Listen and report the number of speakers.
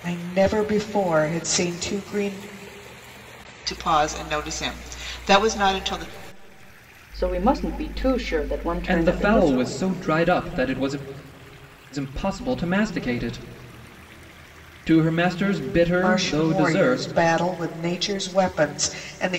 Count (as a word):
four